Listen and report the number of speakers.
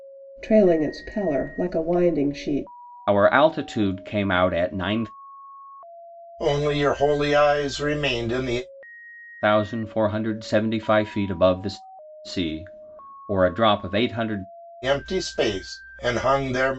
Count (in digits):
3